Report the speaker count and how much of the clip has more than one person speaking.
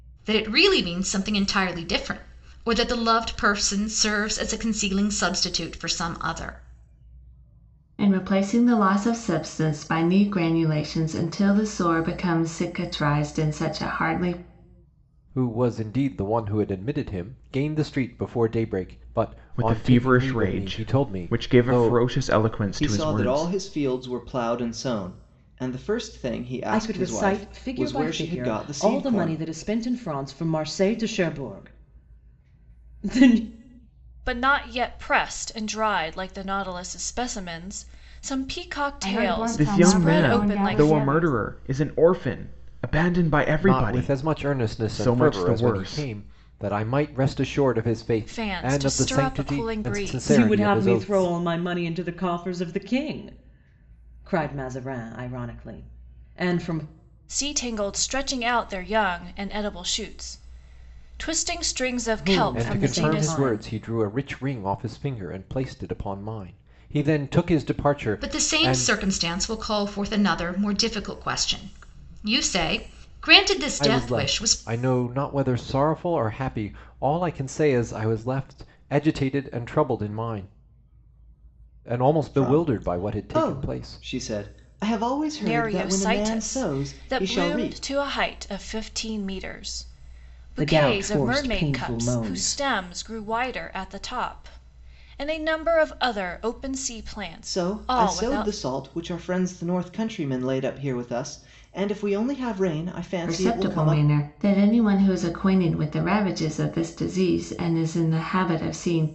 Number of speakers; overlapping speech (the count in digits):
8, about 23%